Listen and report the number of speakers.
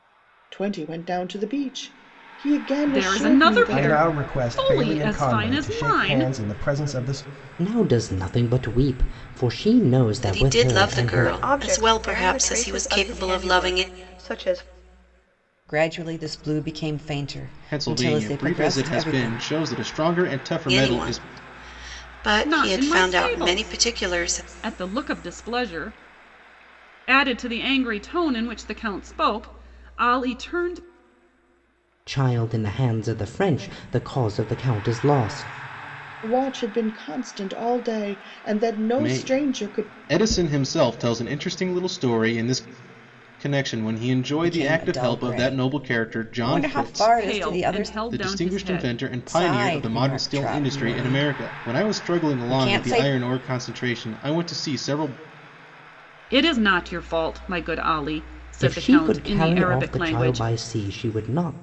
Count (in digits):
8